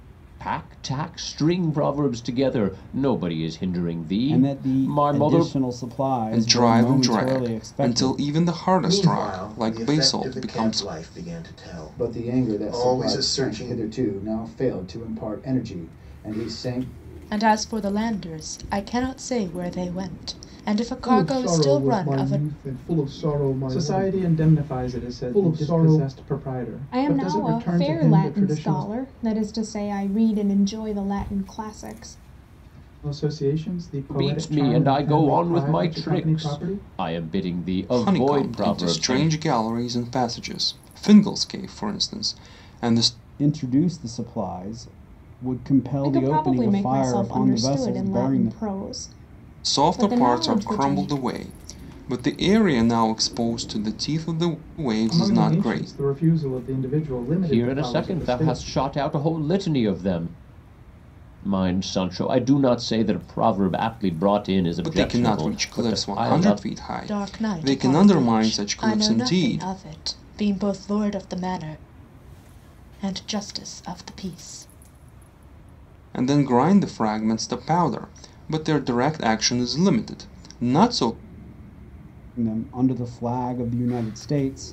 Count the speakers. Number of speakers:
9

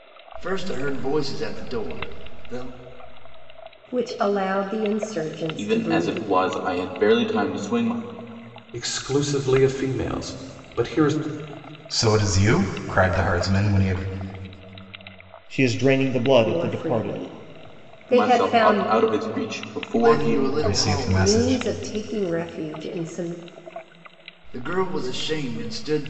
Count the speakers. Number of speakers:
6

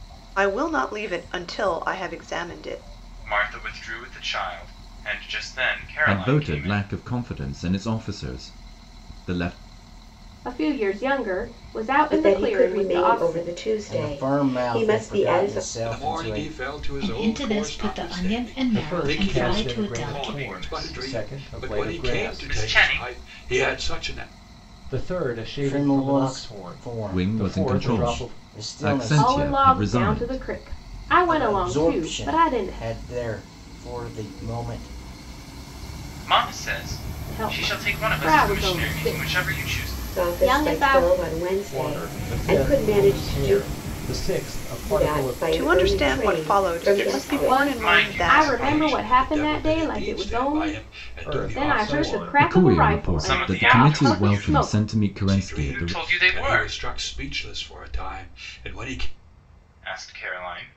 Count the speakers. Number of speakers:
9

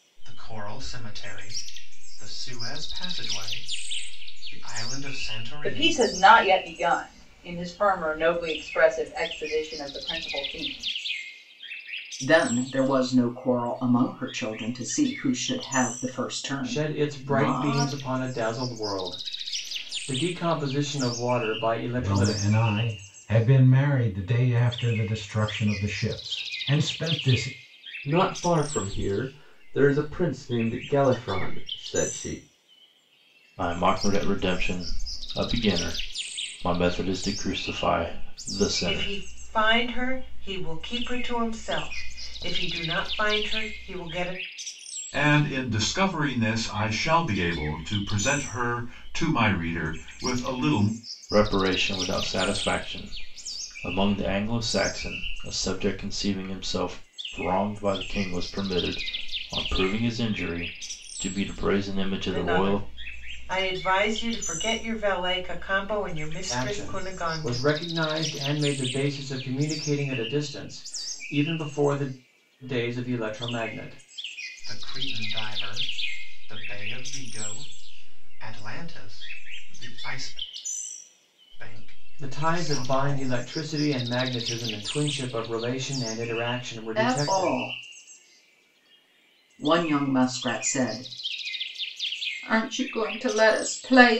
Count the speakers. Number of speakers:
9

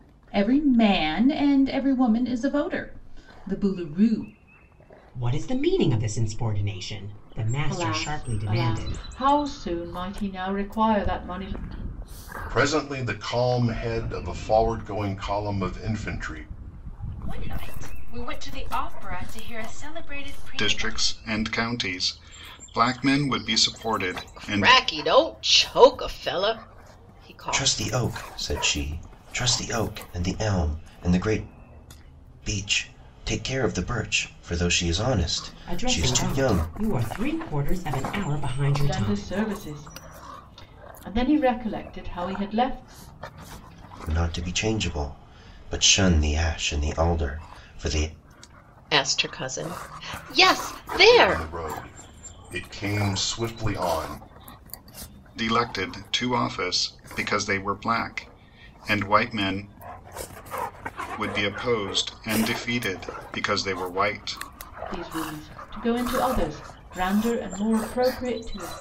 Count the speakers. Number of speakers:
8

